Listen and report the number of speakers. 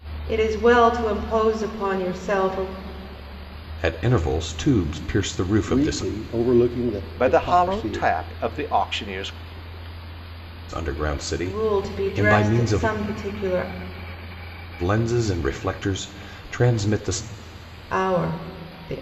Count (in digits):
4